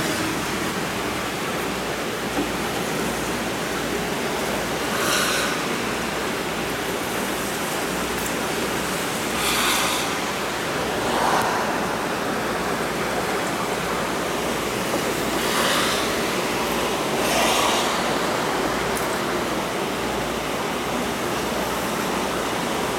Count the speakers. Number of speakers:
0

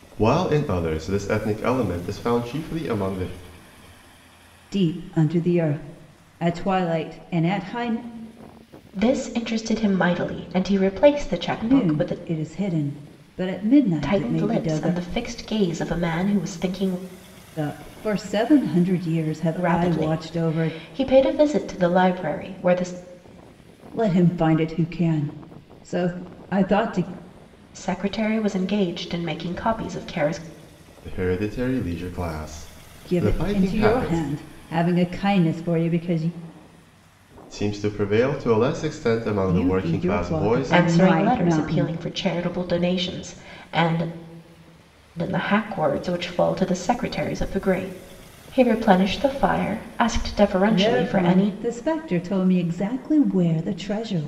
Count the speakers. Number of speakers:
3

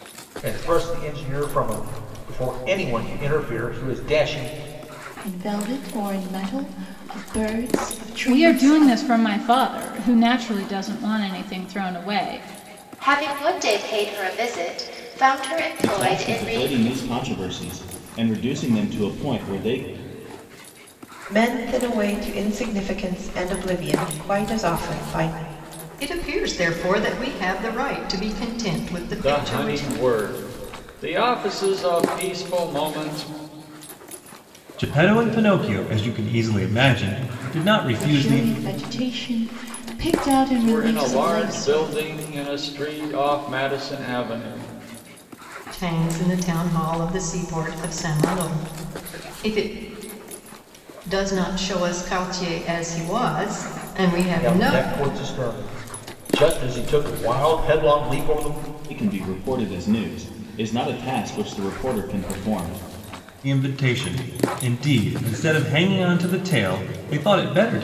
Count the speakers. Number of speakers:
9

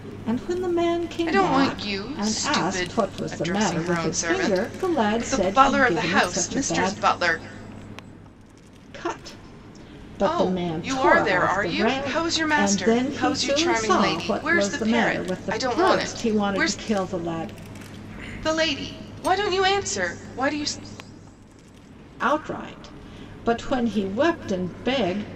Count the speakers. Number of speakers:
2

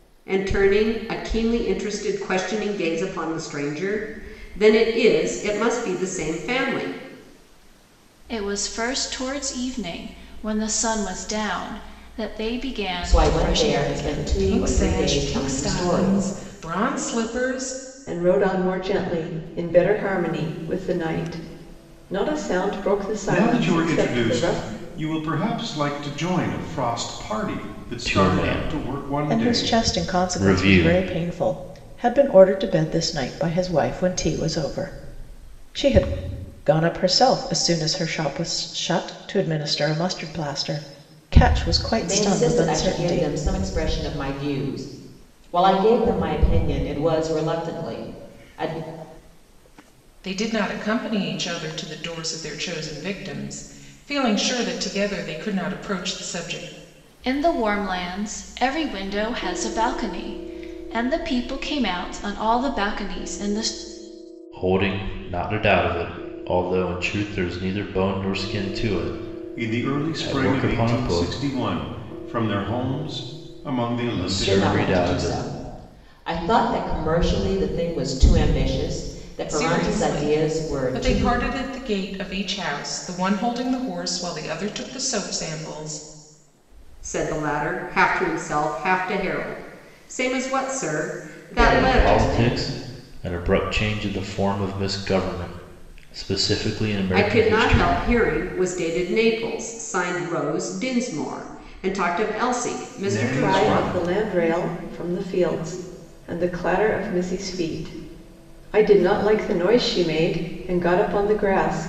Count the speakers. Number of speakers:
8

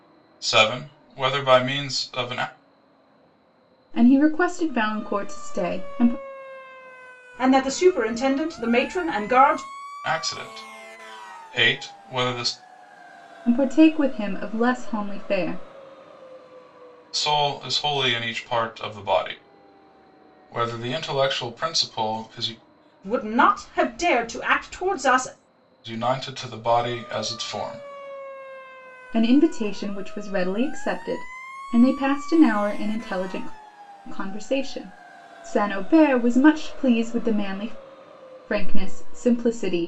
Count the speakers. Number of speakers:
3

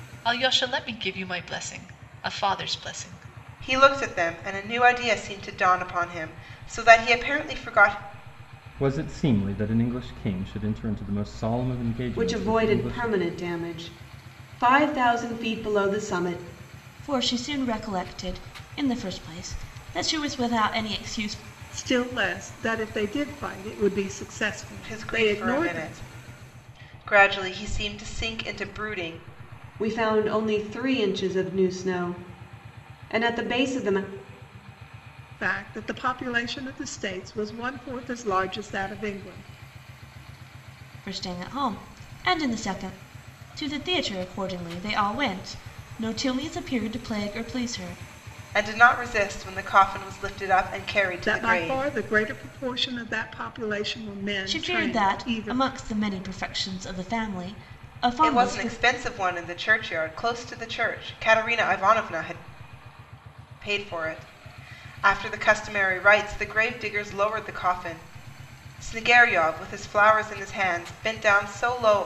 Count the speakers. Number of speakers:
6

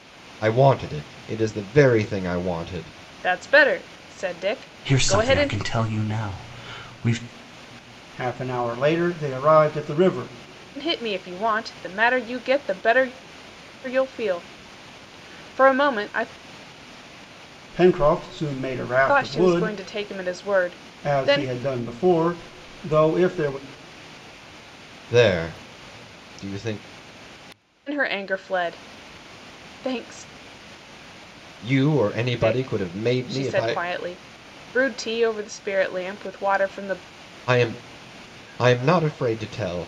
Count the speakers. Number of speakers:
4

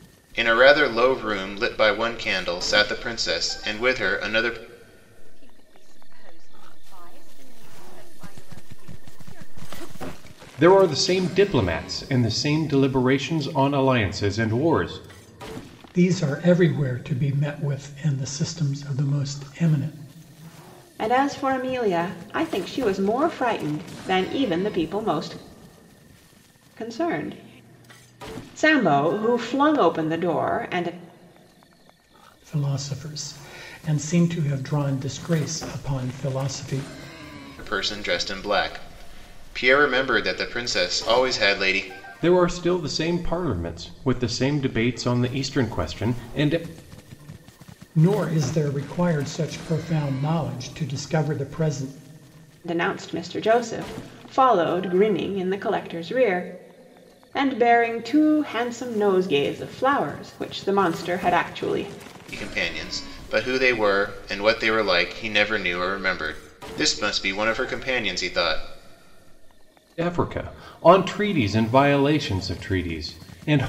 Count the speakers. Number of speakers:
5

